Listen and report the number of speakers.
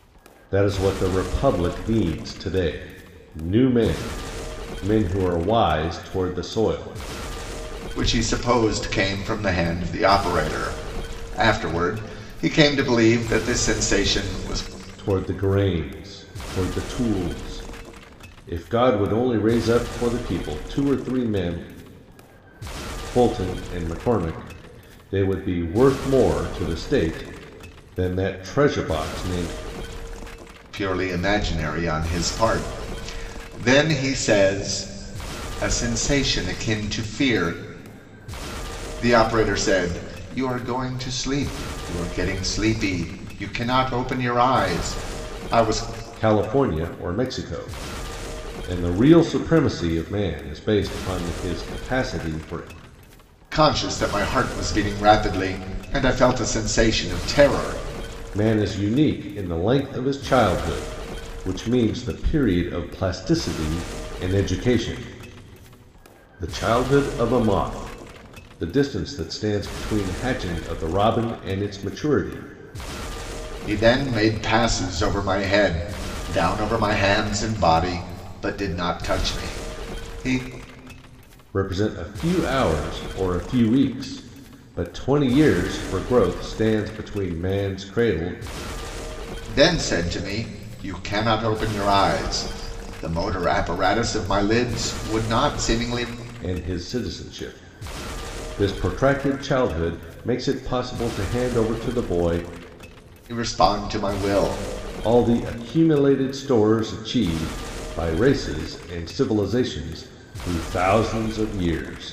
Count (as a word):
two